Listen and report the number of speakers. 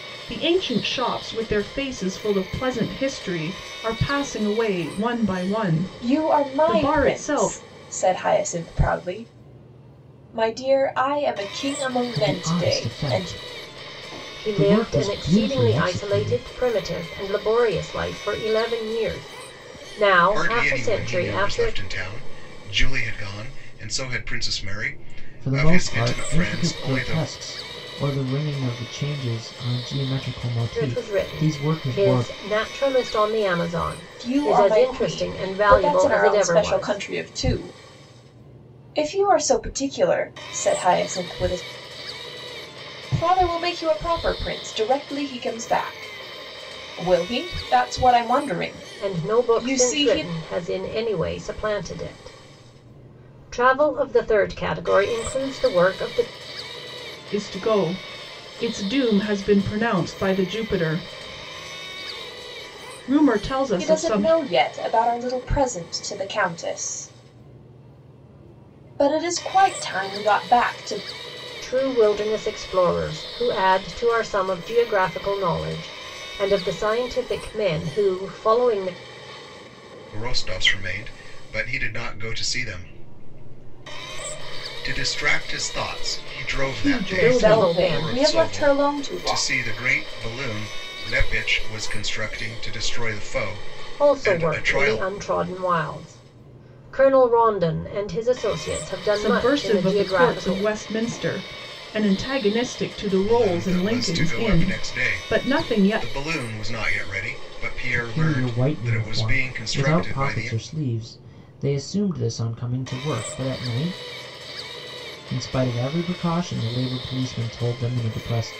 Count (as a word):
five